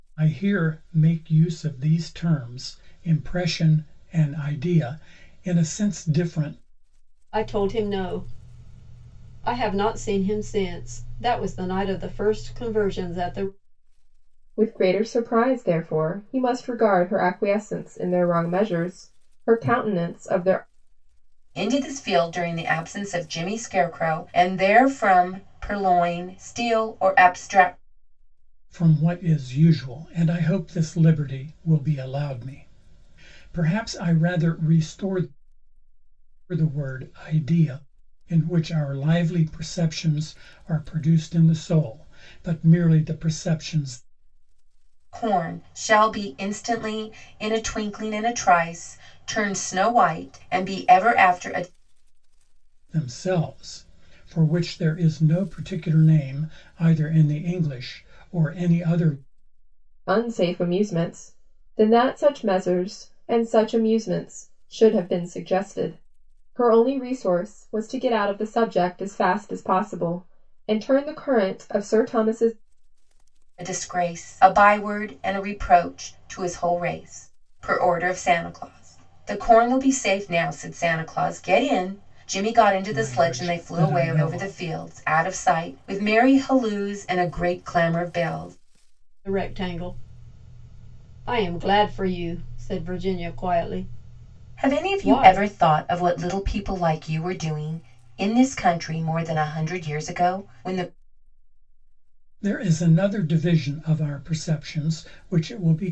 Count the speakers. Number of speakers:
4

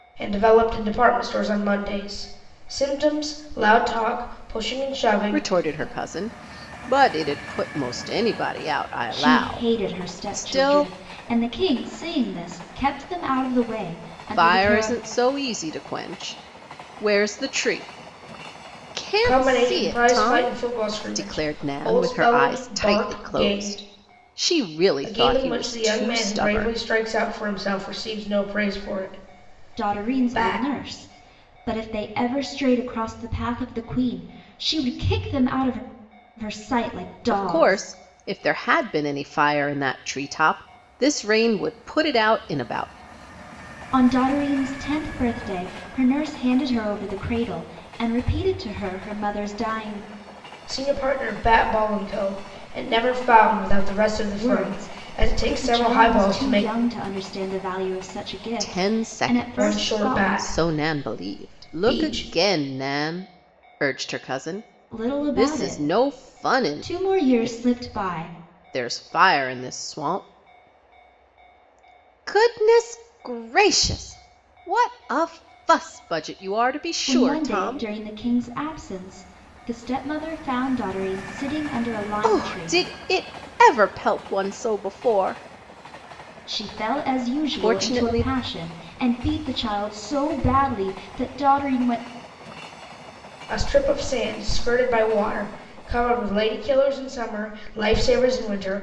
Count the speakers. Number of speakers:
3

